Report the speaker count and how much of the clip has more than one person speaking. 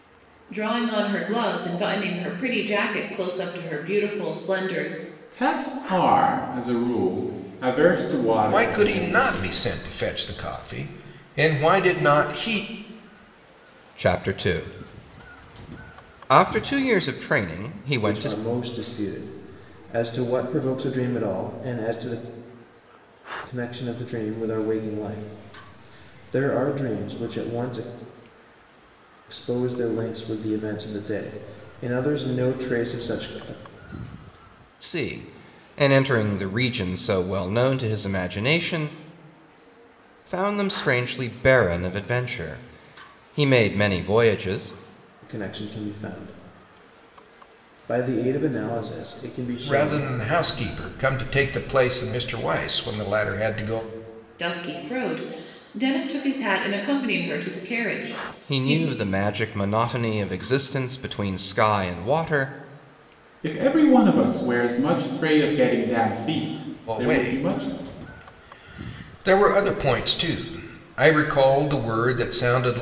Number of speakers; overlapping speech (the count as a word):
five, about 5%